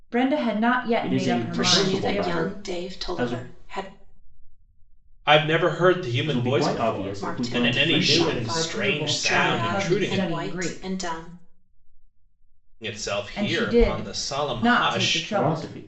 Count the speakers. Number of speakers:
four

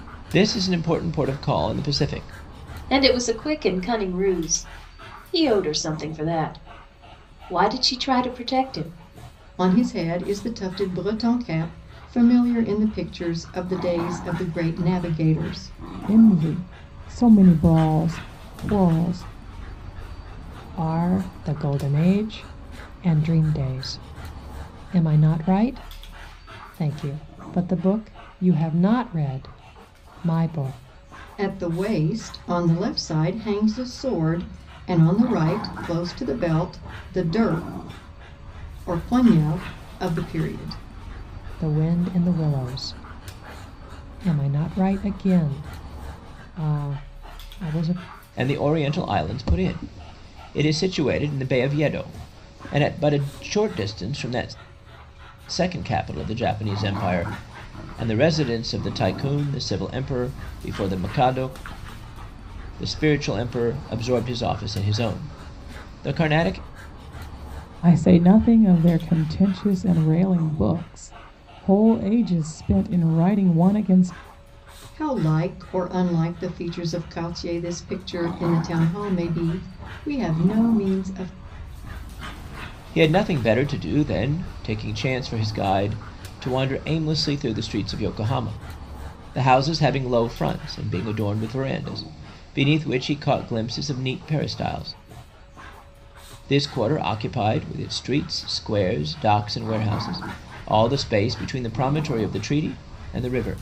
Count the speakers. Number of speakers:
five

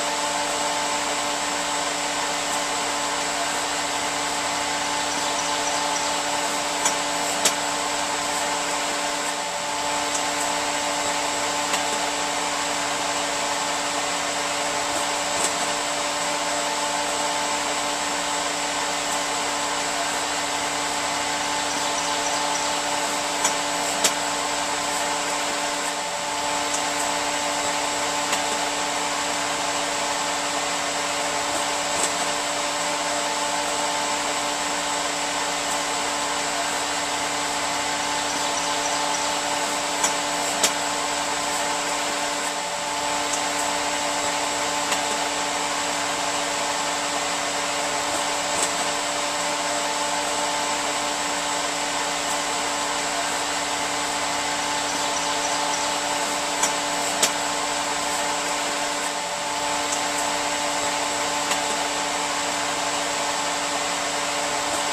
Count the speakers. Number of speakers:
zero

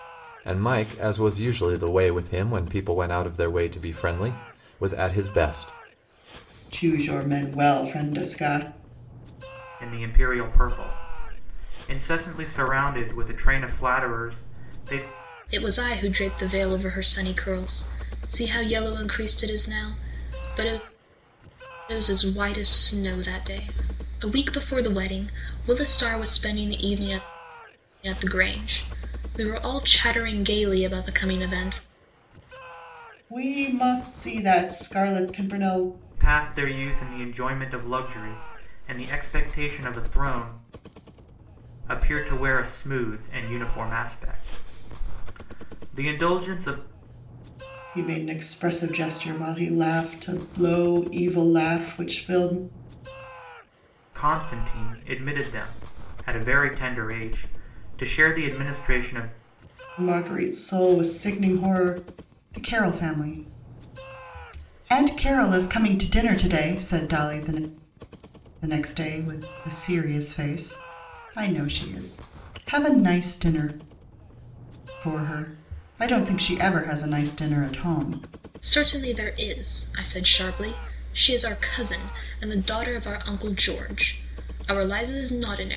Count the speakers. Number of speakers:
four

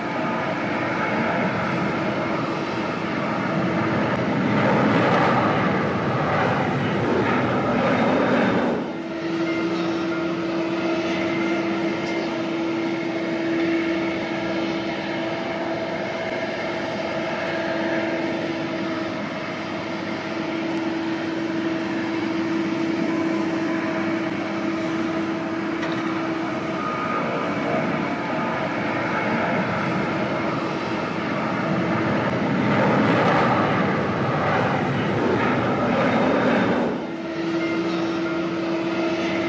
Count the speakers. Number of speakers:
zero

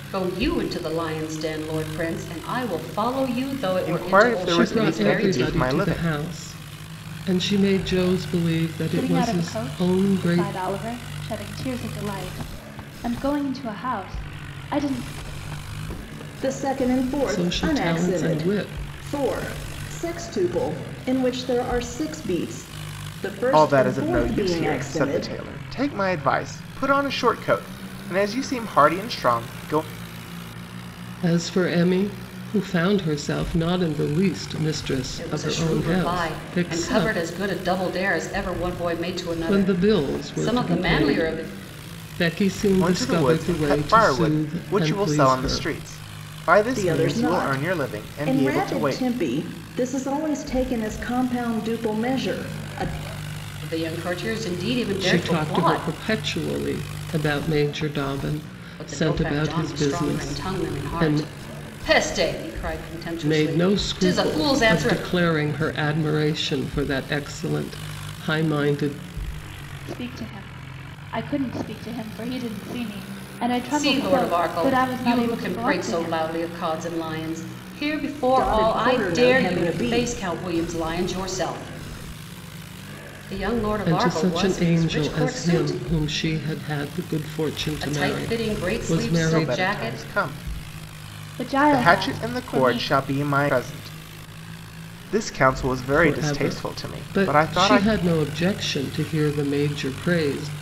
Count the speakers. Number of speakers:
five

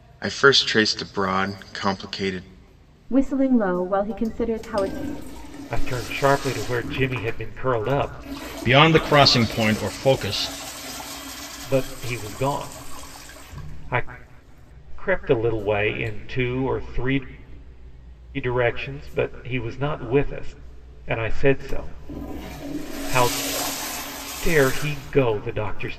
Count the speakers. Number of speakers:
four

